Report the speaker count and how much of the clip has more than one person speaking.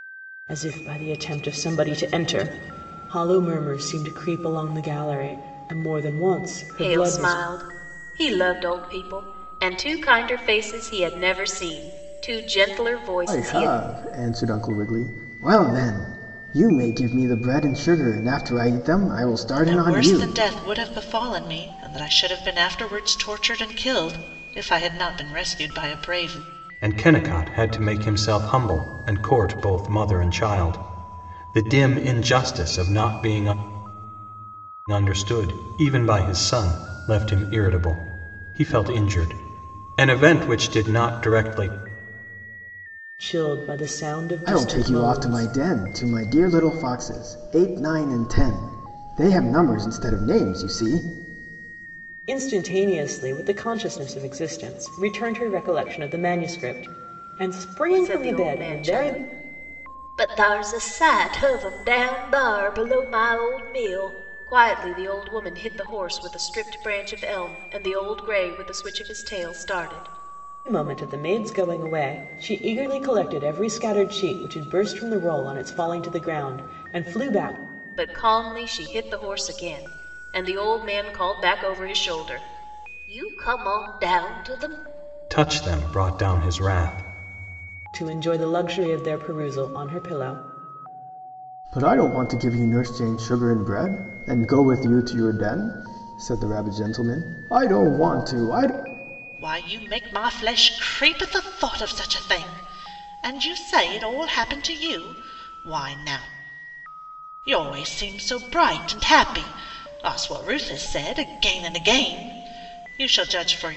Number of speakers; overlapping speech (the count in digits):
5, about 4%